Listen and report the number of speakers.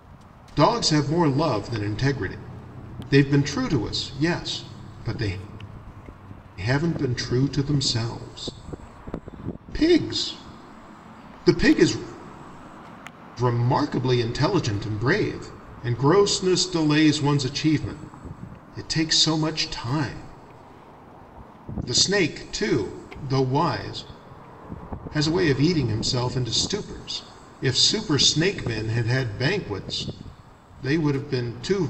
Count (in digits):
1